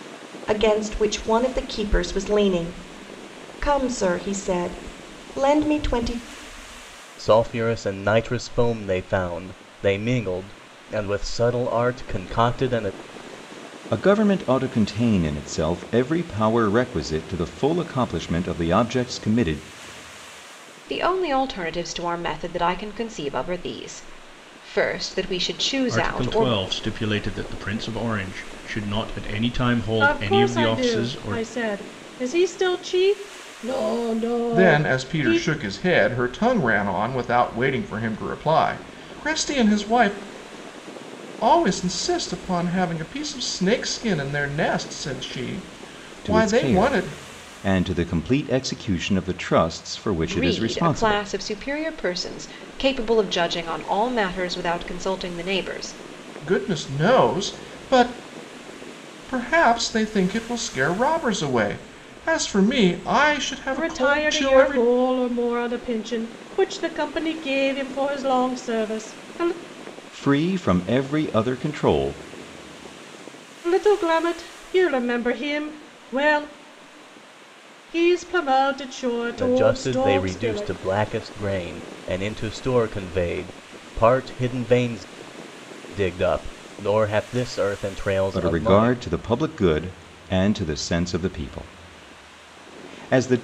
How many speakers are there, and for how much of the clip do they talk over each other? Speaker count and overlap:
7, about 9%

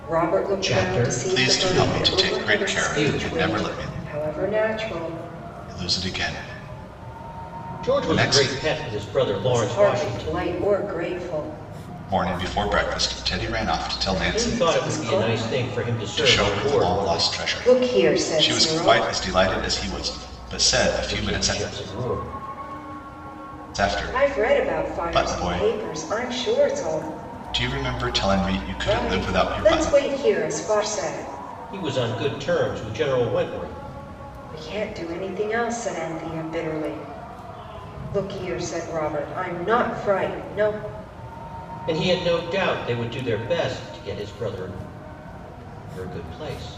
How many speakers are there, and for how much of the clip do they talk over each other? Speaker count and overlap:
3, about 27%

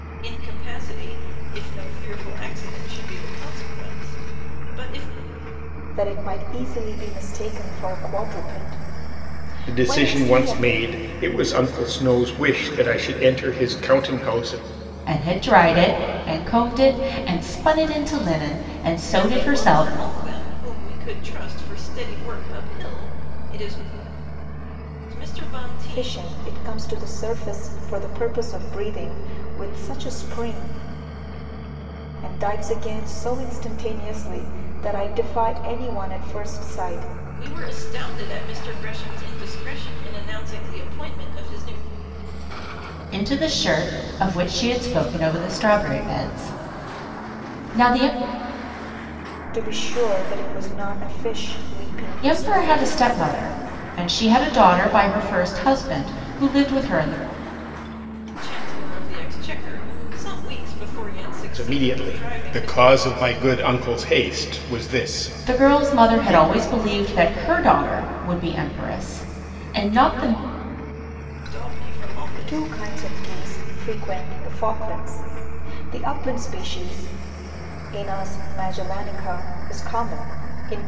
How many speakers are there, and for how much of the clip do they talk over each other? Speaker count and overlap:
4, about 7%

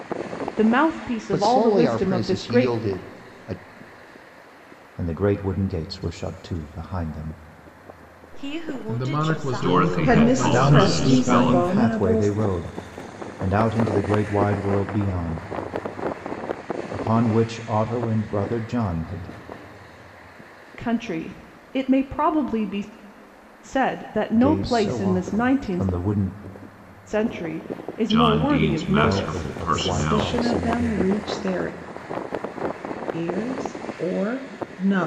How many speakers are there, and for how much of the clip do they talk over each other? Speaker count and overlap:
7, about 28%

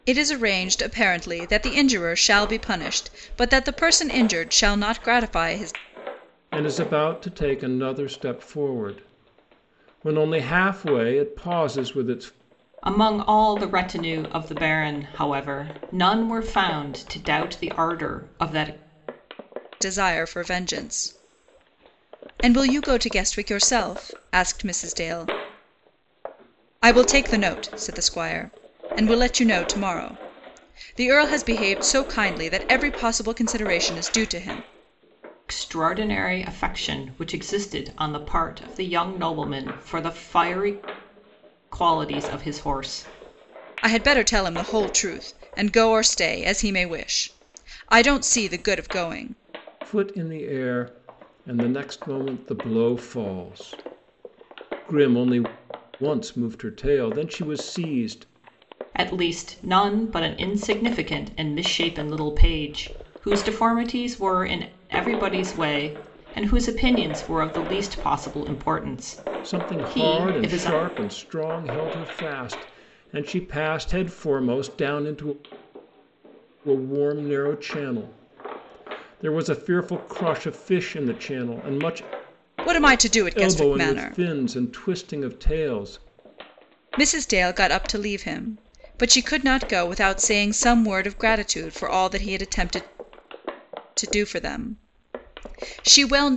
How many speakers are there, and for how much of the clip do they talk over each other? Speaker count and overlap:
3, about 2%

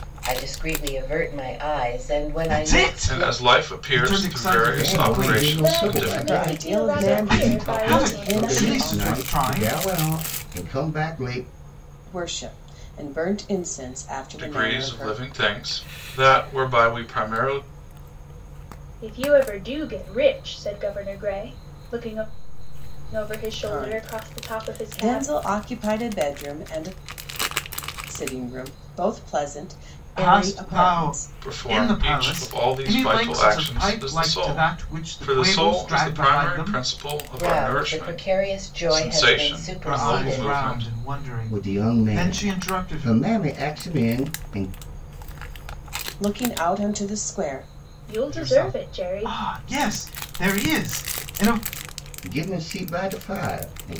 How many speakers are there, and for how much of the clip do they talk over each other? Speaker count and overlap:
6, about 40%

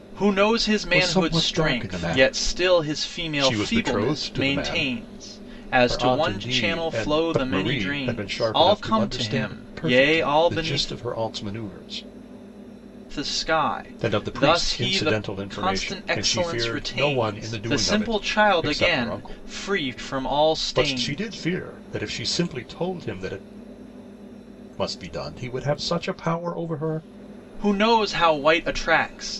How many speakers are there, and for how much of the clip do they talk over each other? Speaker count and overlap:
2, about 51%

